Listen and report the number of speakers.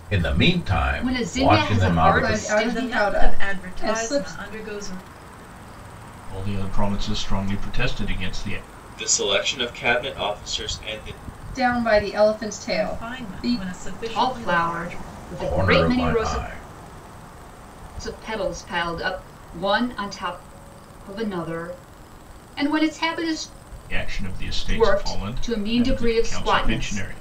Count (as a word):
six